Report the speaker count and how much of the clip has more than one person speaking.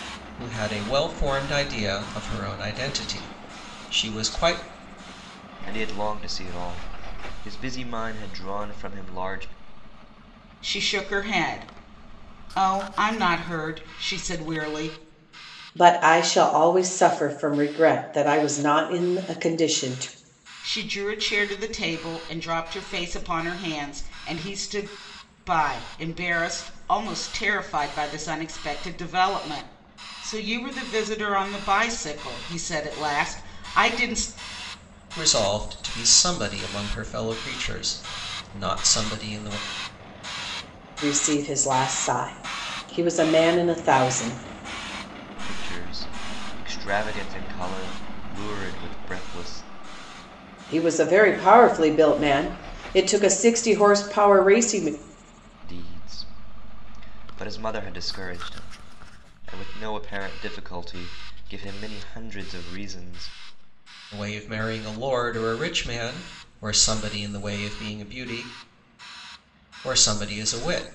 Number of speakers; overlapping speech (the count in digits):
4, no overlap